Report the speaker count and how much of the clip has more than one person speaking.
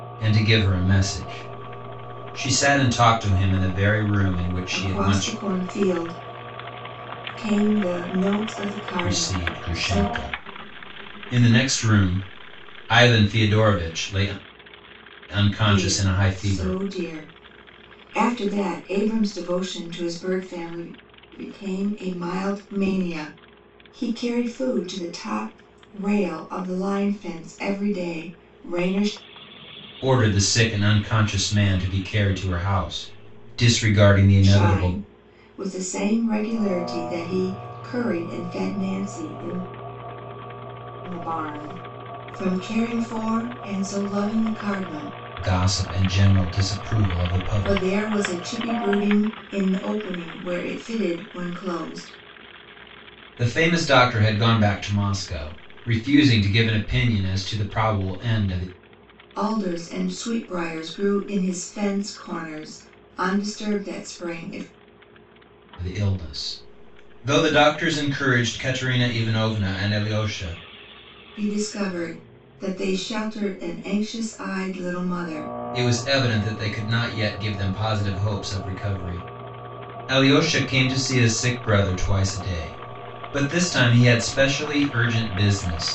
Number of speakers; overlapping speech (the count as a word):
two, about 5%